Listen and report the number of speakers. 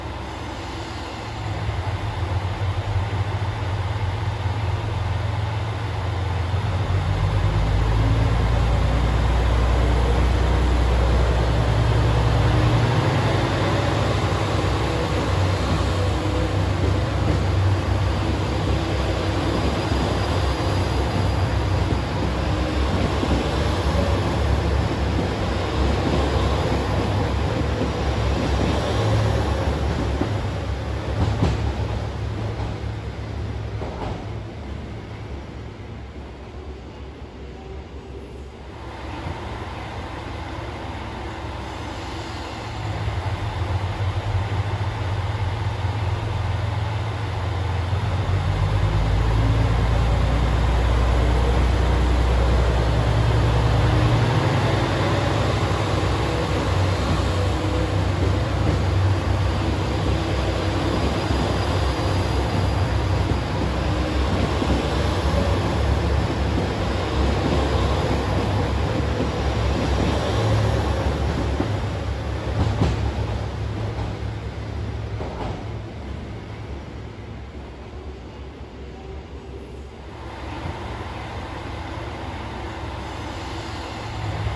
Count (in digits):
0